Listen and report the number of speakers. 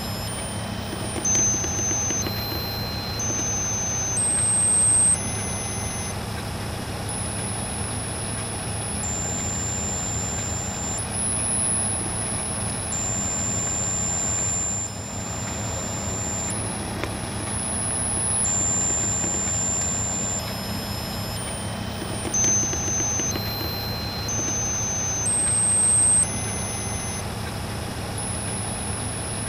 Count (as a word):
zero